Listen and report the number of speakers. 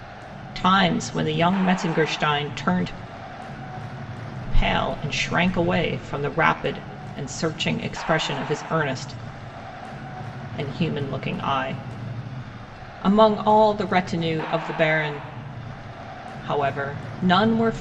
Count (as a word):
one